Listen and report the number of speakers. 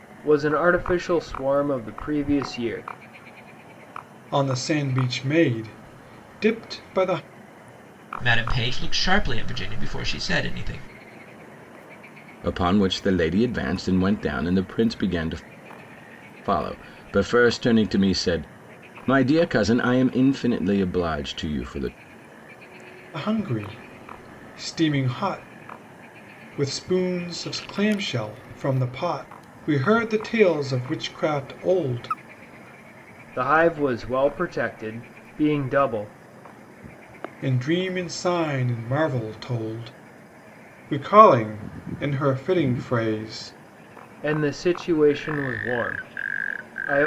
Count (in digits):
4